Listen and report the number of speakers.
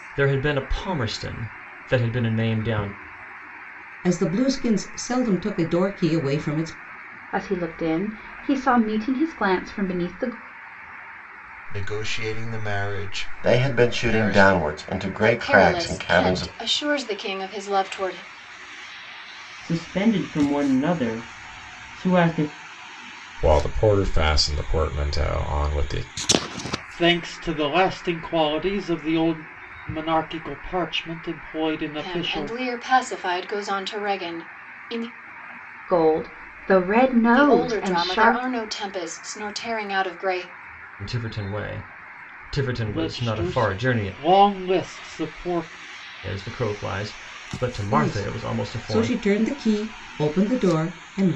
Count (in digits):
9